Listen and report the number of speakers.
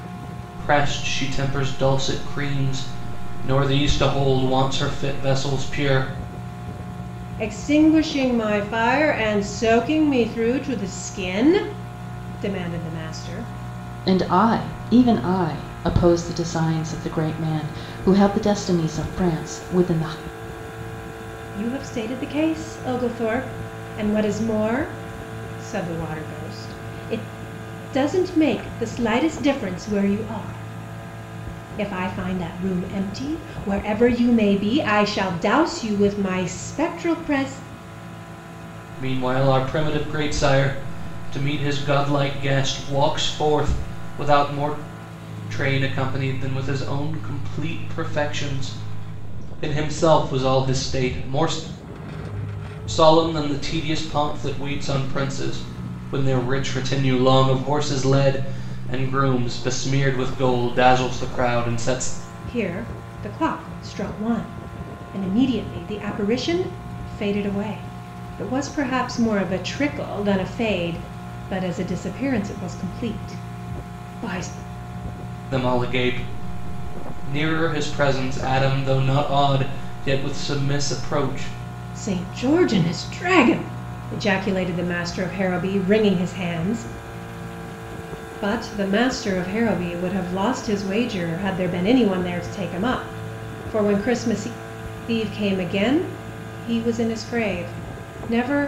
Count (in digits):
3